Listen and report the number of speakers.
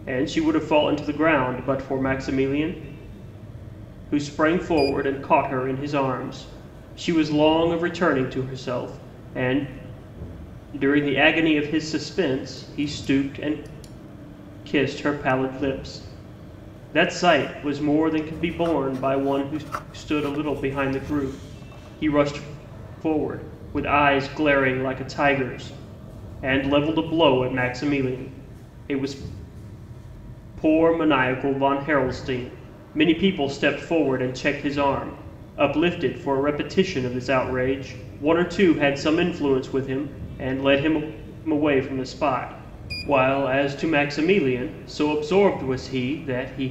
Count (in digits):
1